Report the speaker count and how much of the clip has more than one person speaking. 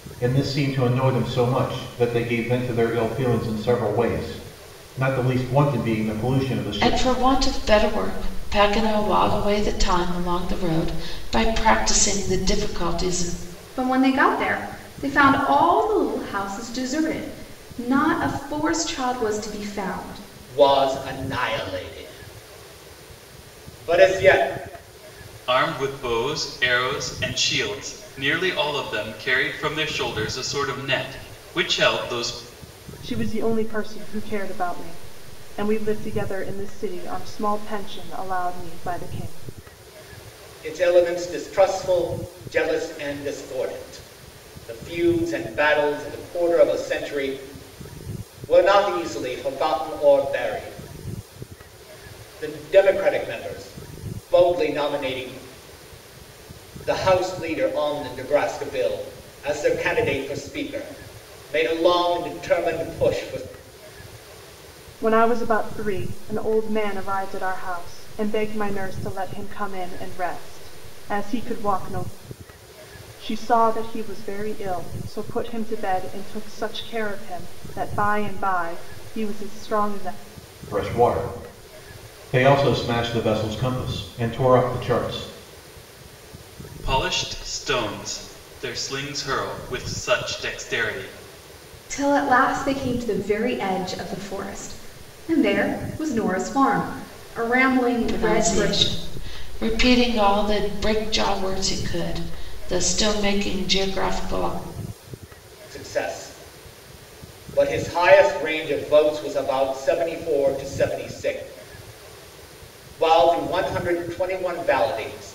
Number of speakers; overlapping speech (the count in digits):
6, about 1%